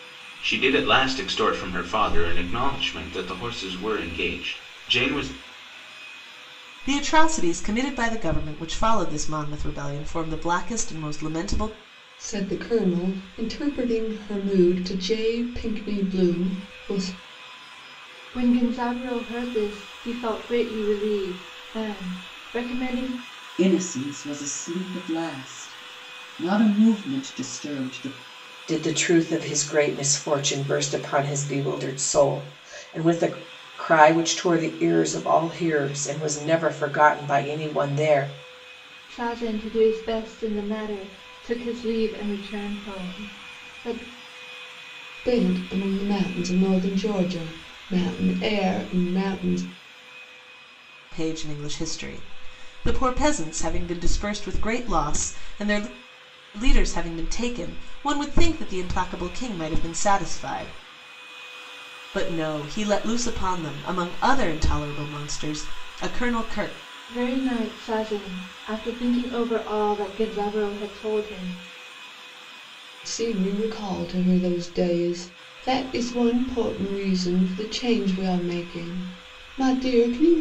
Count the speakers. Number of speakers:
6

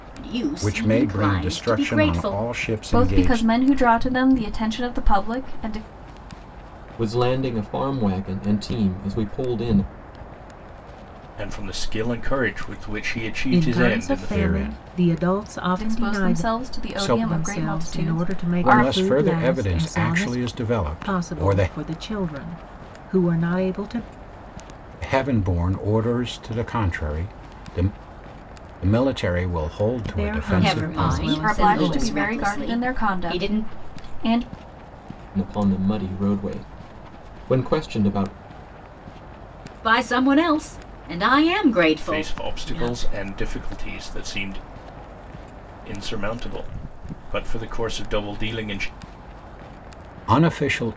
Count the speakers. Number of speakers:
6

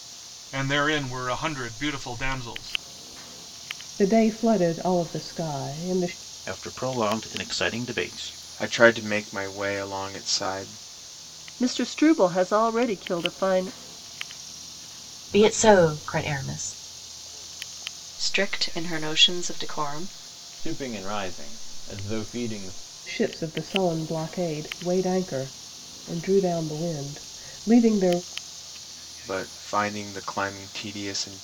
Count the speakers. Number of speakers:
8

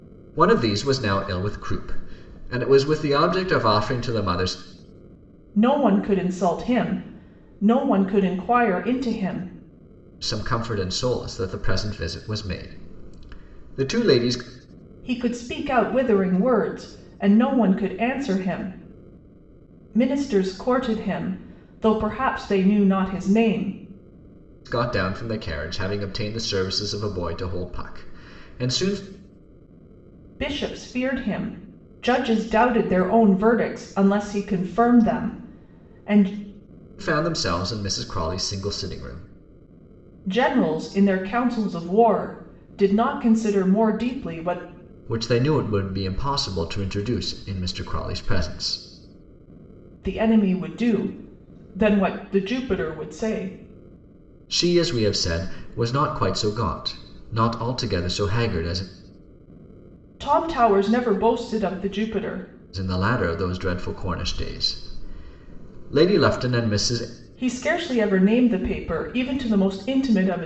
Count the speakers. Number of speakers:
2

